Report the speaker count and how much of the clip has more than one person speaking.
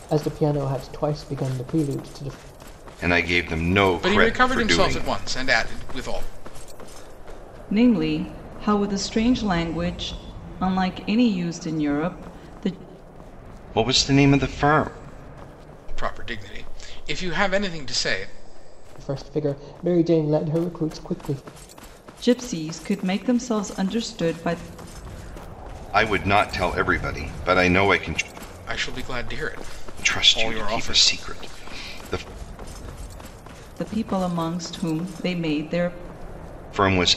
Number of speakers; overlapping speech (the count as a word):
four, about 6%